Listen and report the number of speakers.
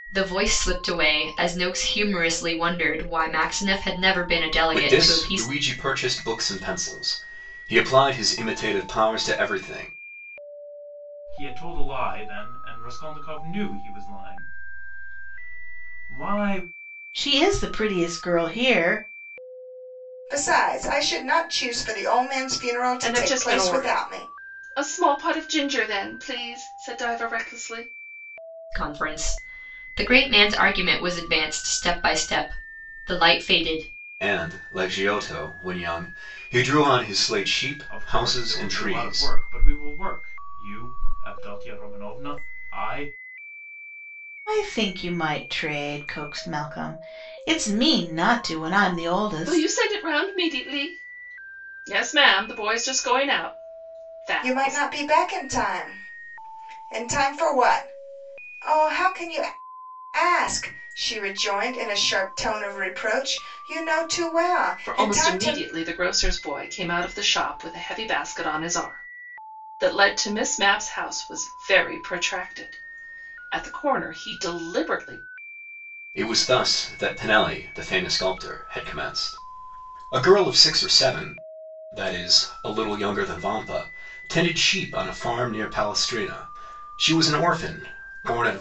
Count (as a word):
six